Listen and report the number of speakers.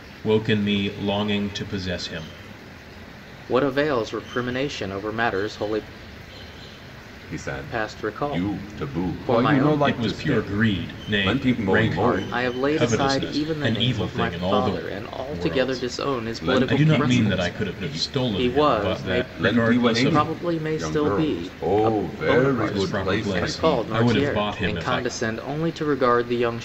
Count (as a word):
three